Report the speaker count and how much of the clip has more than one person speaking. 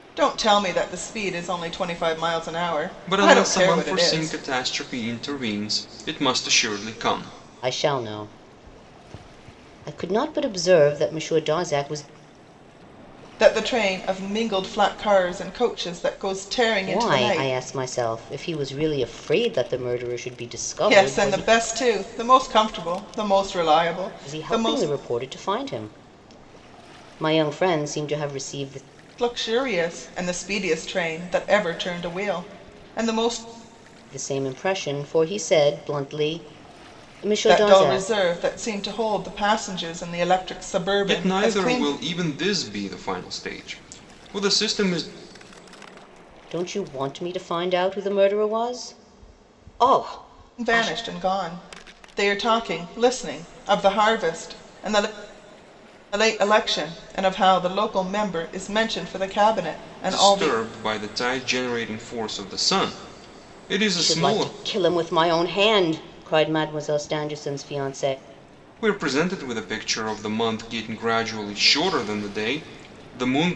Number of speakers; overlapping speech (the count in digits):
3, about 9%